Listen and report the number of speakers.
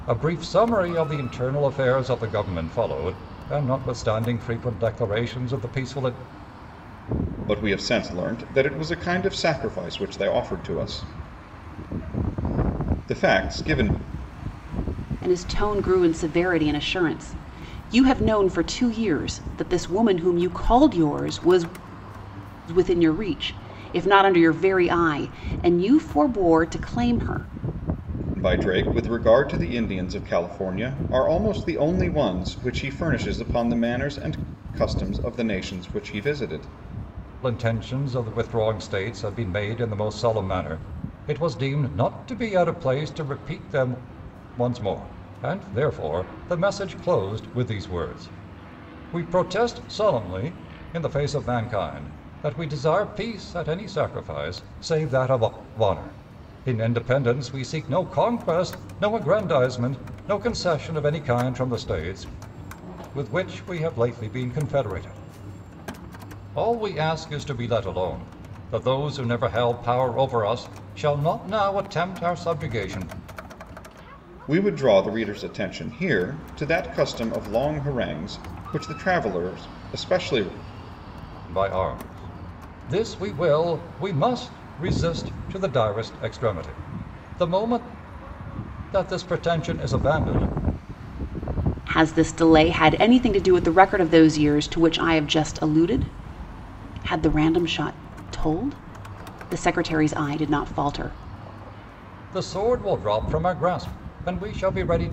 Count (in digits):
3